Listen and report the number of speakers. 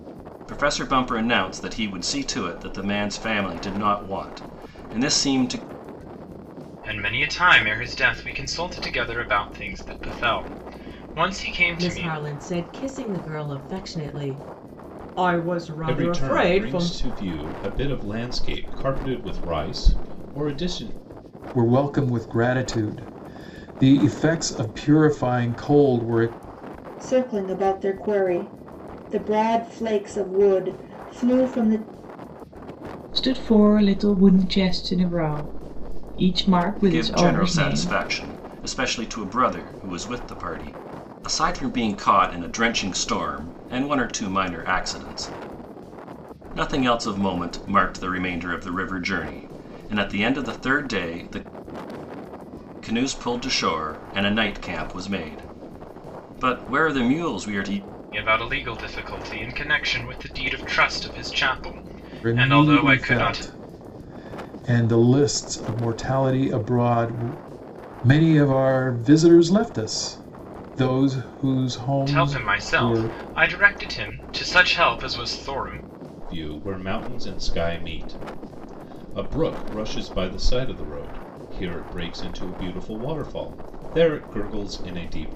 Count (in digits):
7